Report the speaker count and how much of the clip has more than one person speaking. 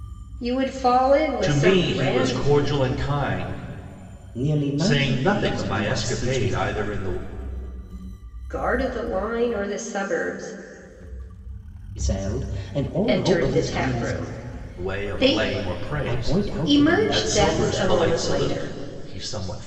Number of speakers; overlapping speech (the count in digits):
3, about 39%